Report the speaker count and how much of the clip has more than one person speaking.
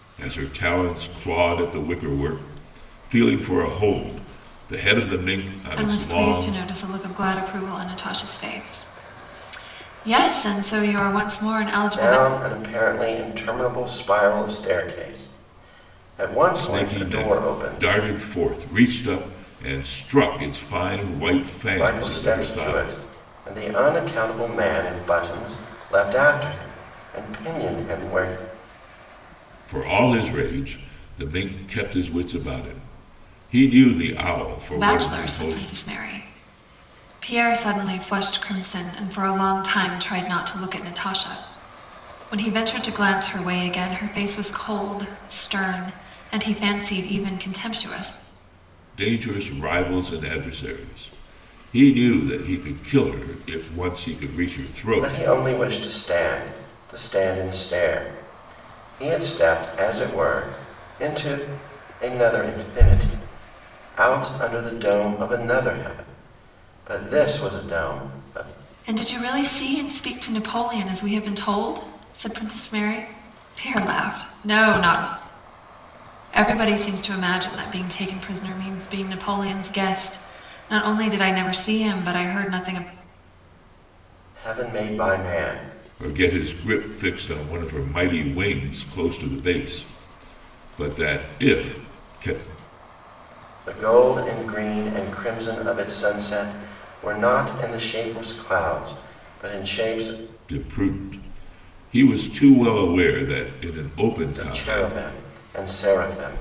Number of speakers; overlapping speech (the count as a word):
three, about 6%